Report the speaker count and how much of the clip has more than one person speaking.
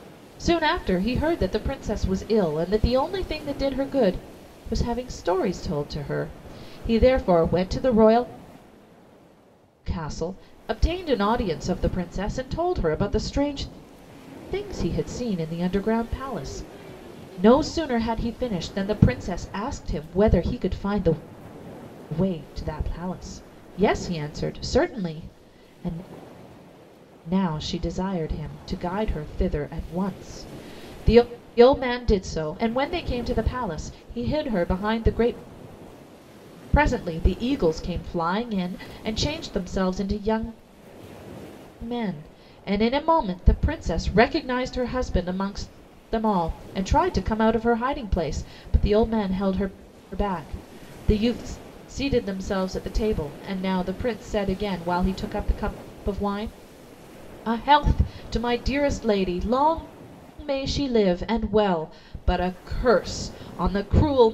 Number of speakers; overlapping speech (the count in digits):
1, no overlap